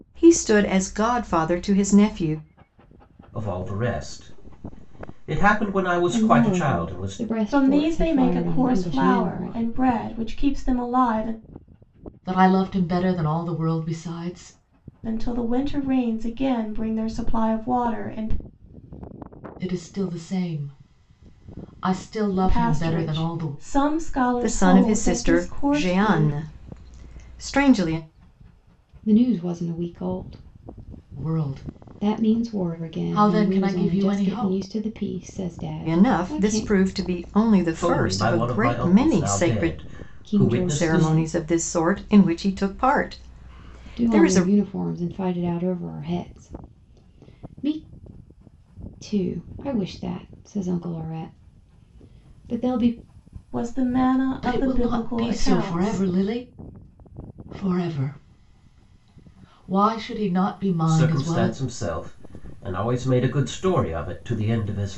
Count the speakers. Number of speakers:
five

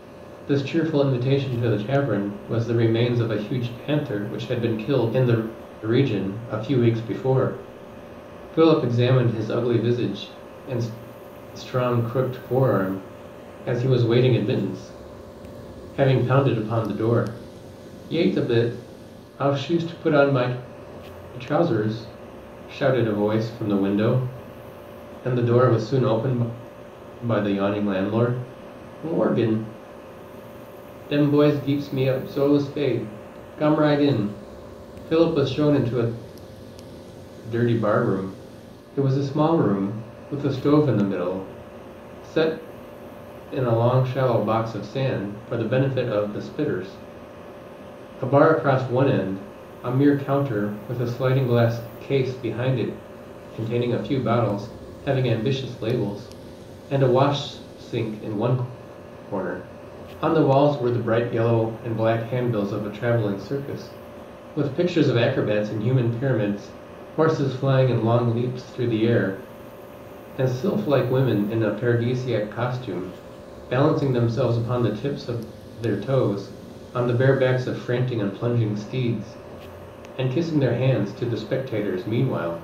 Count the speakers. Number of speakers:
one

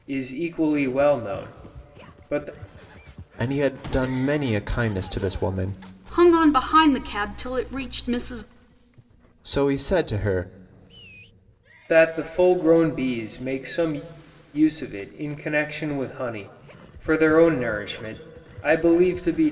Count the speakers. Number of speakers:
three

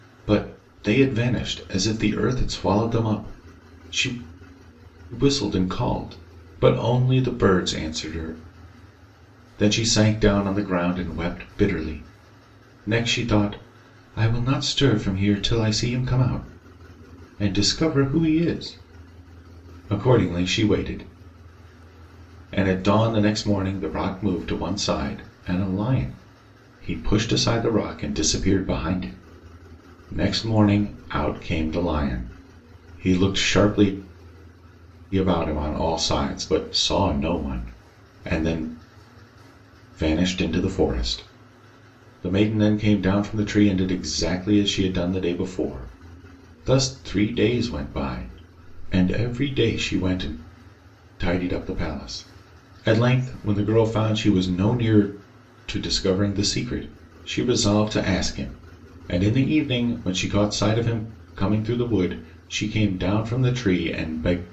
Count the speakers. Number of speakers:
one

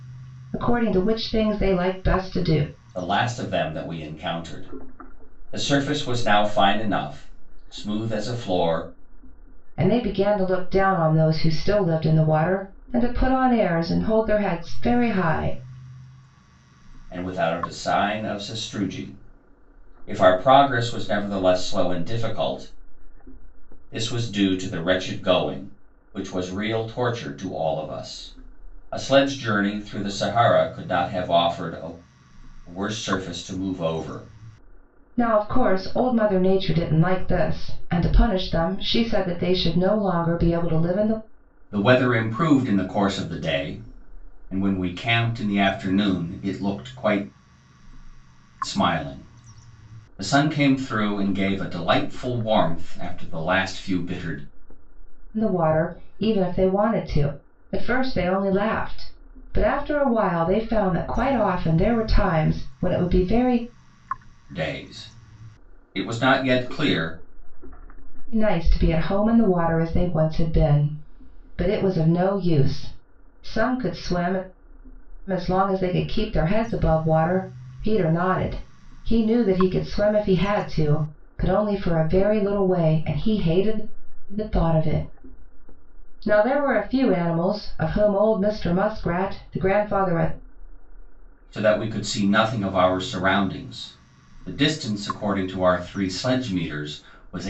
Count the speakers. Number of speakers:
two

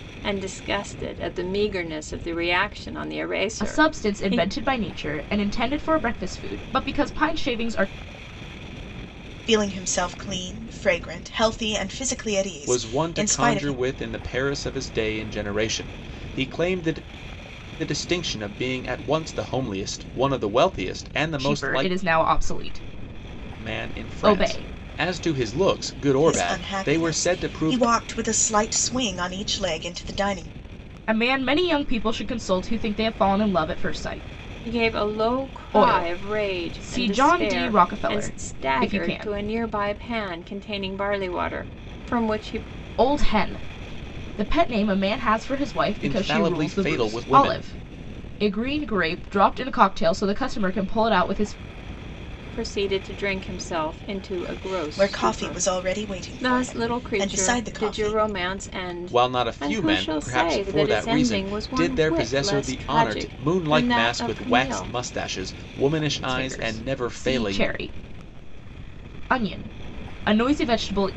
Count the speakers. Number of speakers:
four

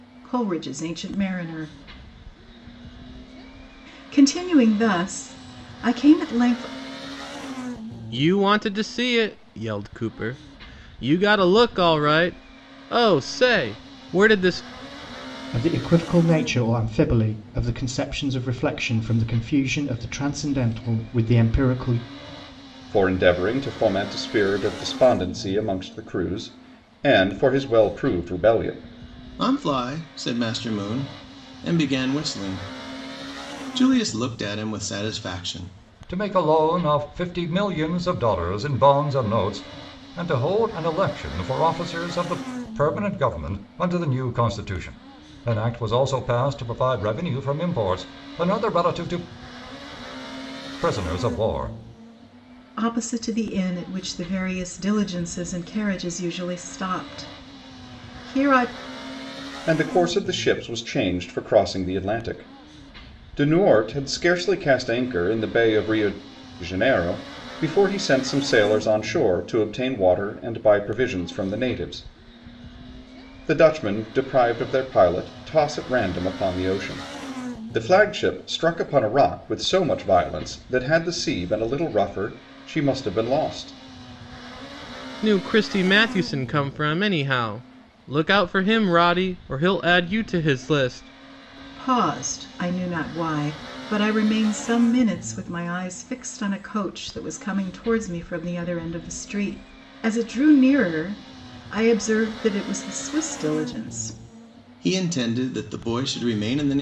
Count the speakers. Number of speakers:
six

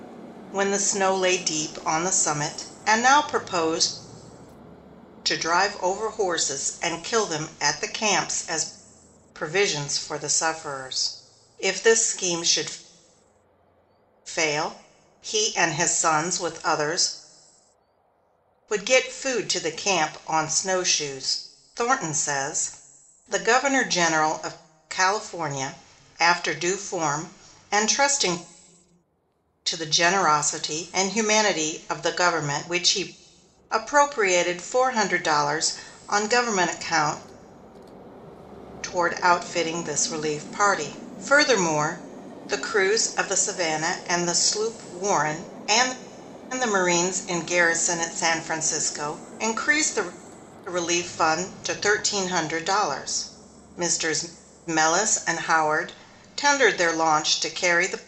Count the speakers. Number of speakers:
one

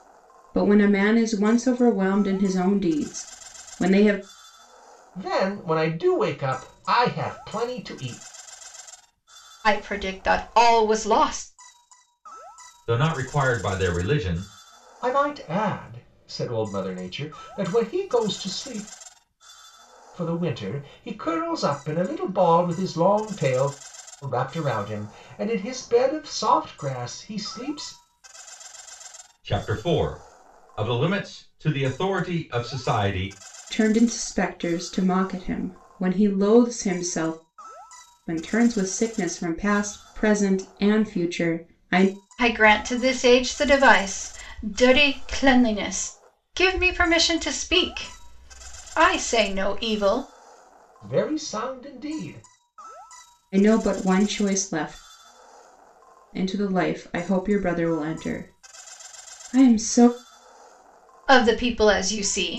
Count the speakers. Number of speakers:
four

